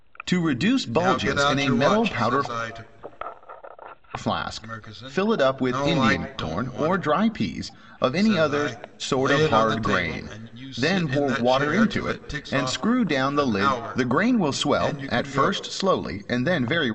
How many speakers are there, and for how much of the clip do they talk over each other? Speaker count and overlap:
2, about 63%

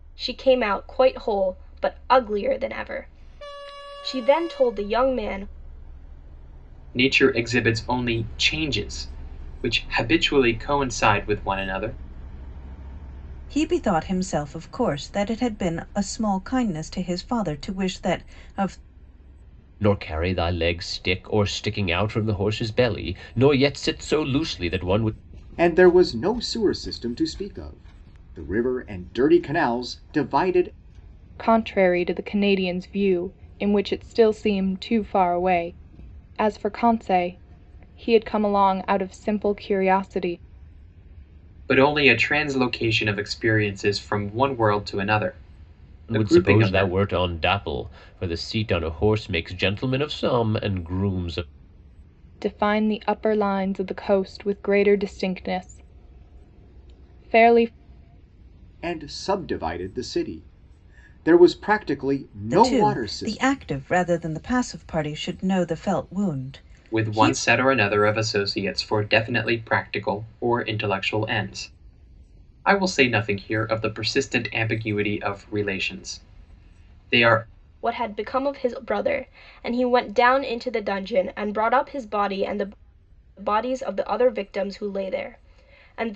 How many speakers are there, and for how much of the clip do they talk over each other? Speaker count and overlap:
6, about 3%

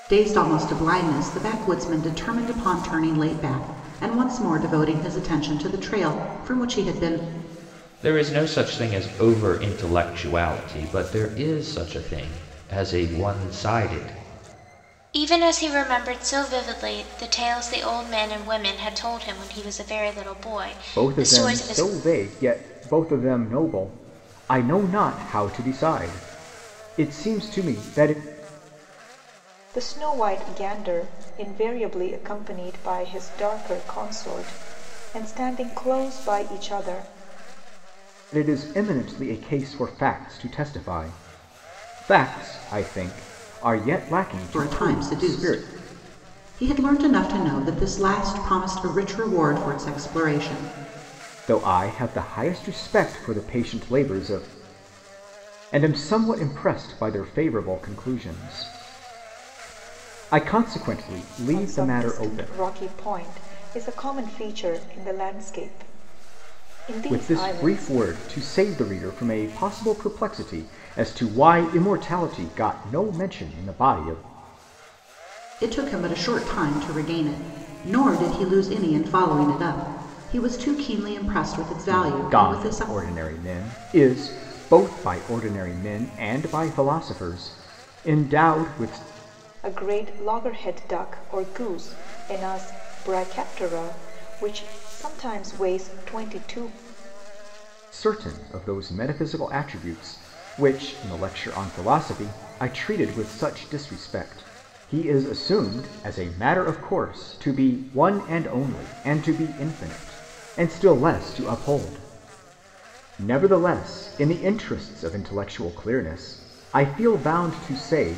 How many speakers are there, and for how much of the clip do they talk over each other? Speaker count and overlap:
5, about 5%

